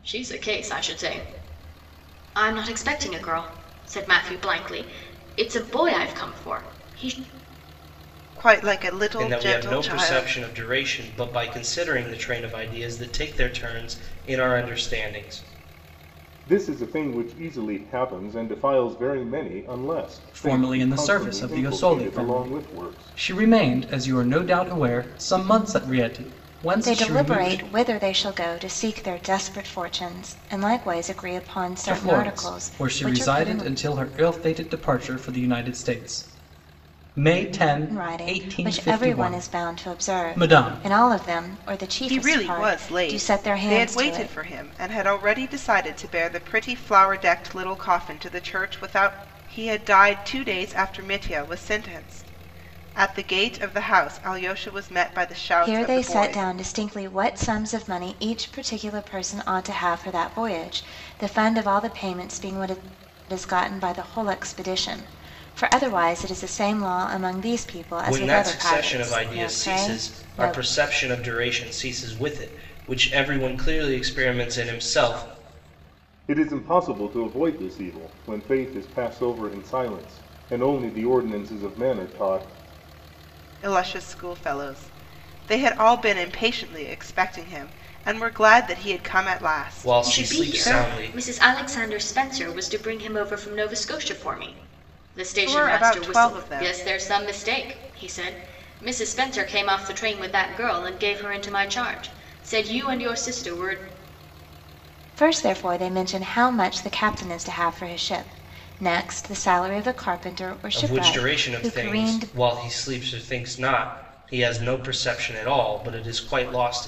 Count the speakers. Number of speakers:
6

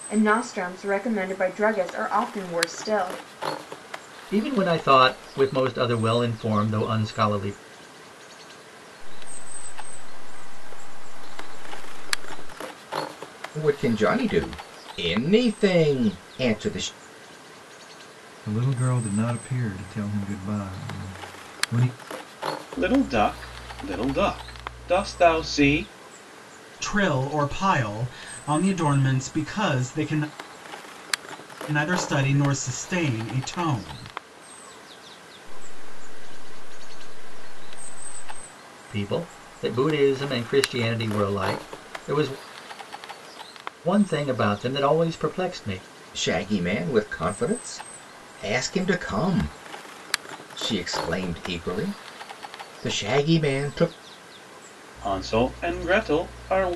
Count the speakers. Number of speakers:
7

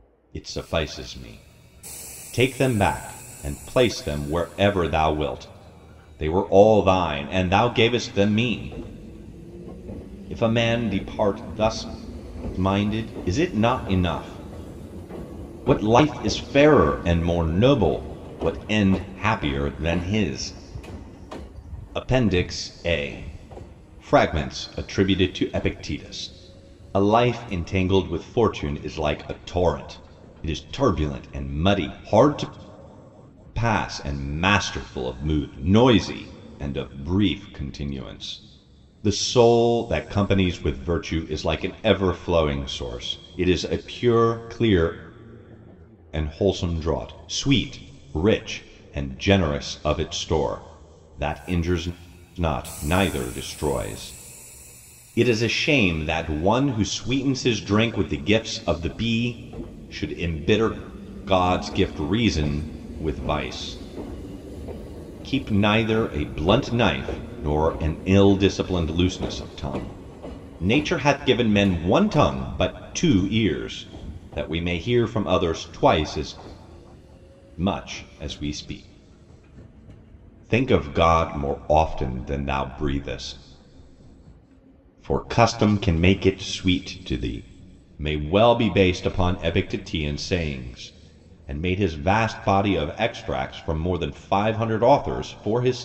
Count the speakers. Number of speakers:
1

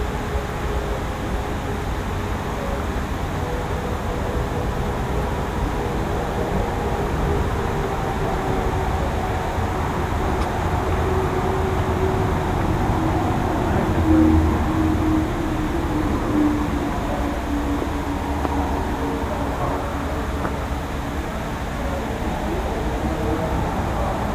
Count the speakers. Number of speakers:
0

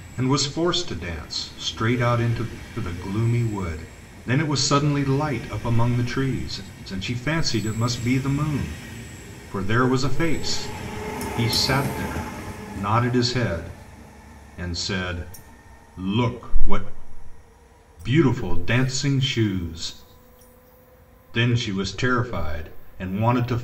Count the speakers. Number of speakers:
1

